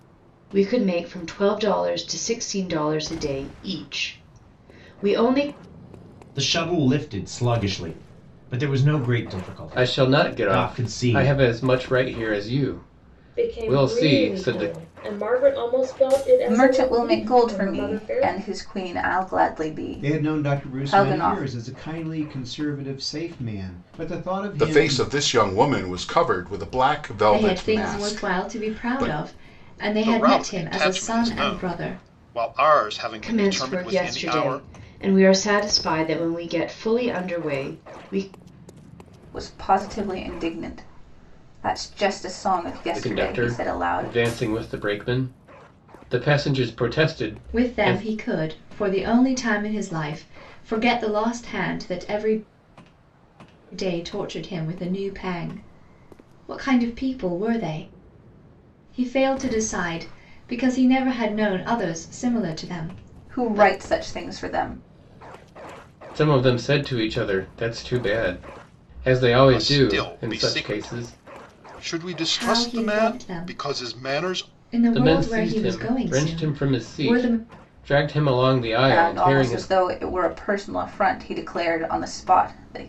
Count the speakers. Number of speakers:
9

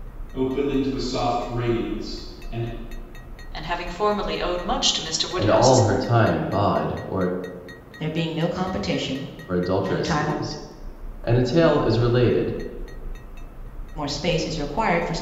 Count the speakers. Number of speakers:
4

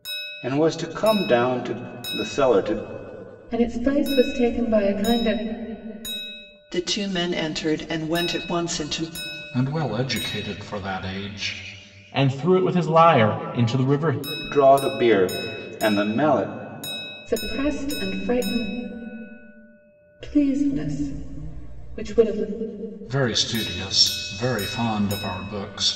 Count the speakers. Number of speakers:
5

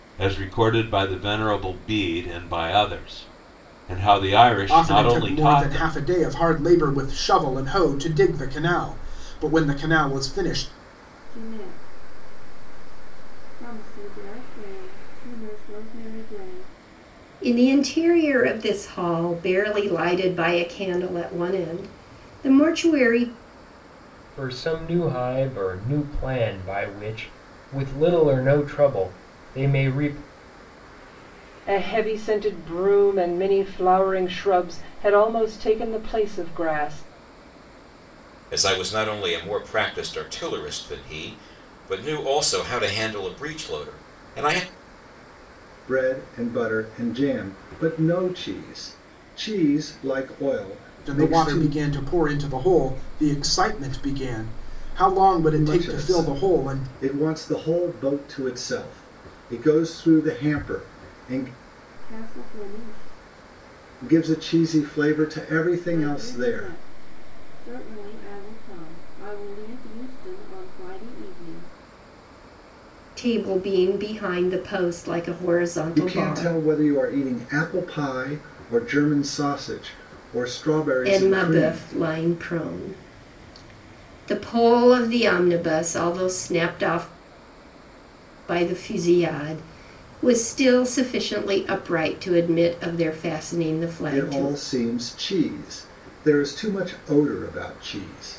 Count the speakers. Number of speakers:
8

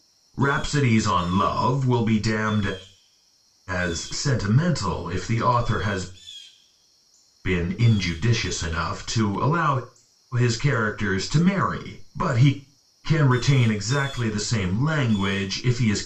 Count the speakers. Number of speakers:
1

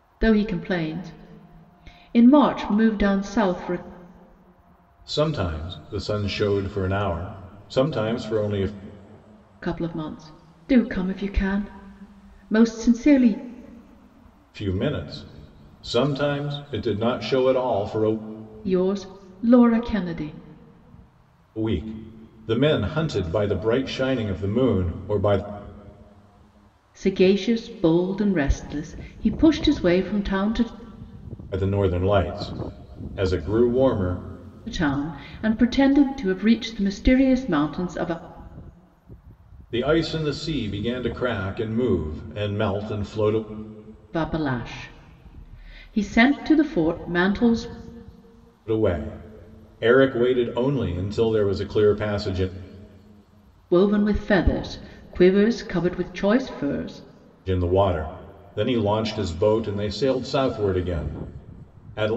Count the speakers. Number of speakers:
2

